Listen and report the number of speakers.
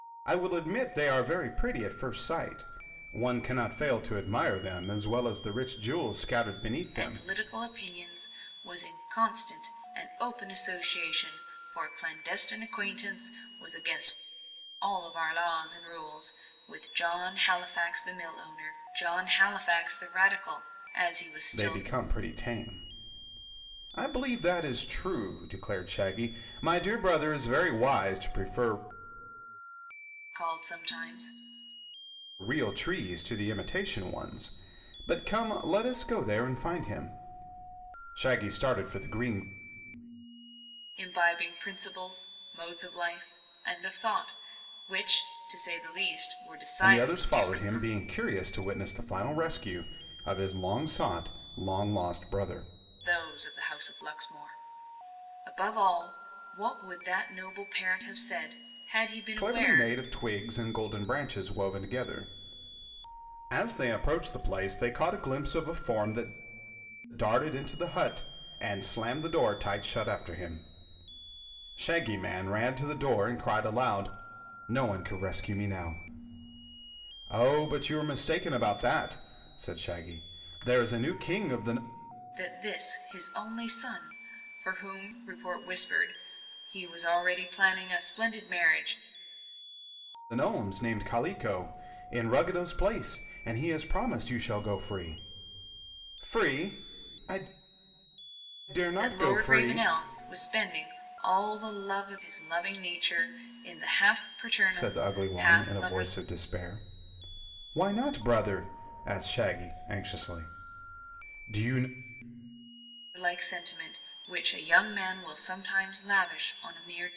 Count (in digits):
2